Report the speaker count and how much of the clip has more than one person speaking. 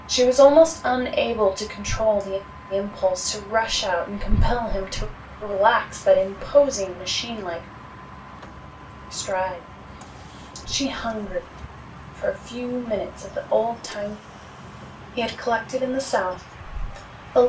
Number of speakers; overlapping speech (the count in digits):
1, no overlap